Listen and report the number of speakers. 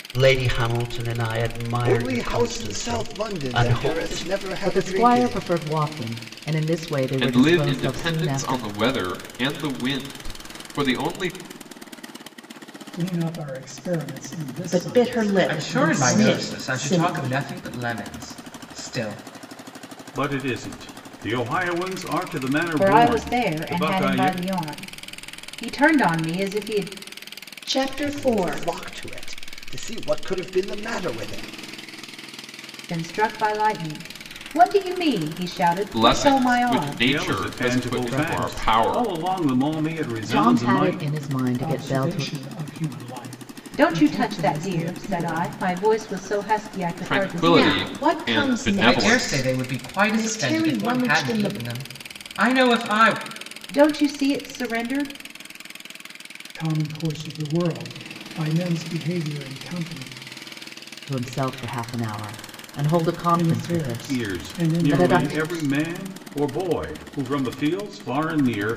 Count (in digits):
9